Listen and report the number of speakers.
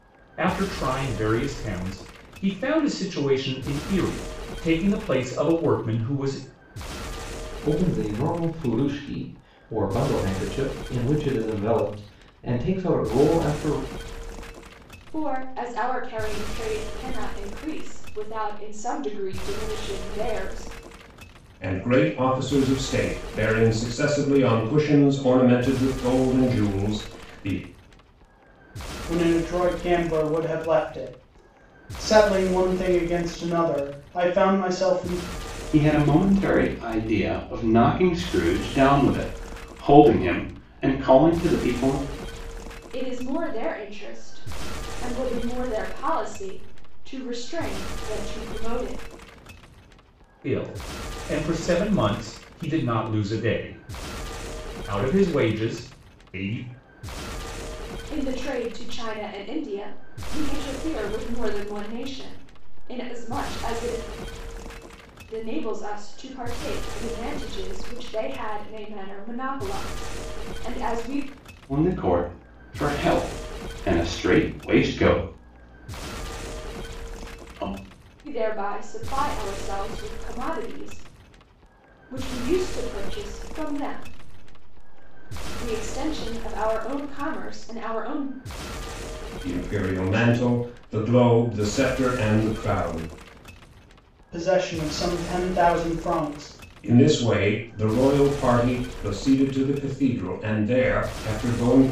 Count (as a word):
six